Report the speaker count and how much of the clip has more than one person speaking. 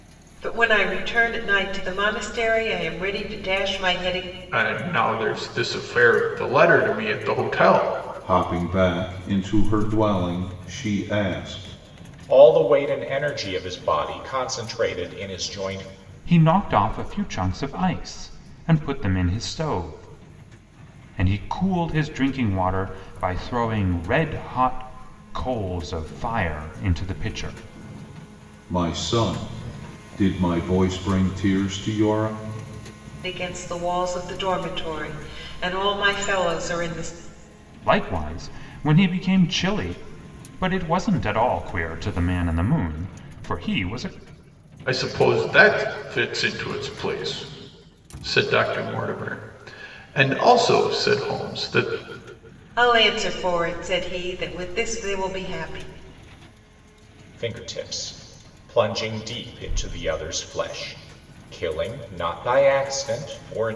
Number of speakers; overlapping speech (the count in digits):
5, no overlap